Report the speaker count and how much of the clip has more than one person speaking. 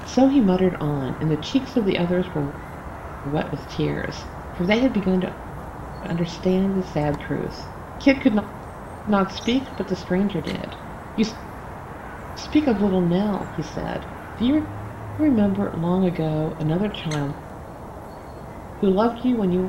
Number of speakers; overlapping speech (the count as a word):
one, no overlap